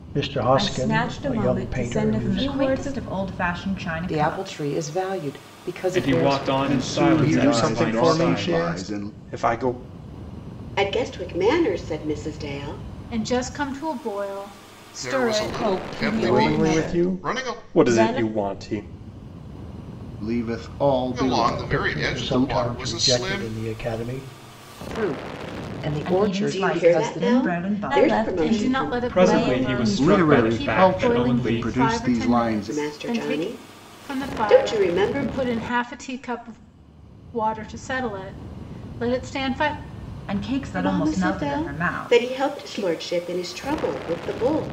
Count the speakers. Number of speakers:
10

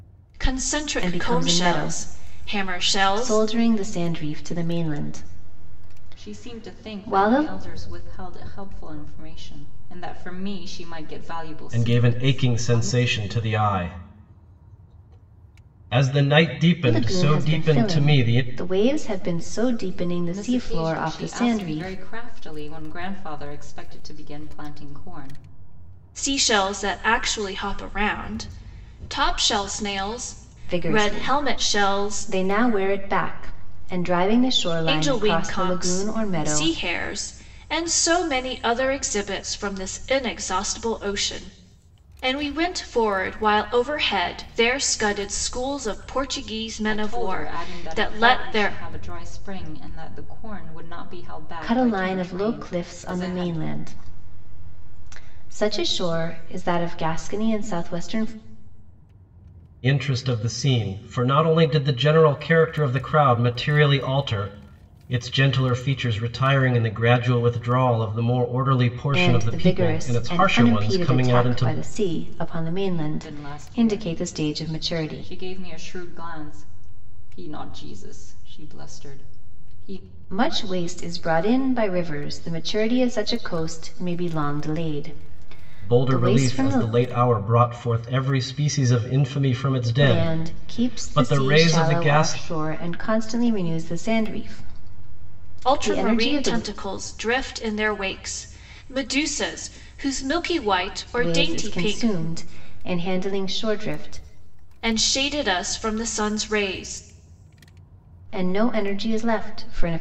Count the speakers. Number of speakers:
4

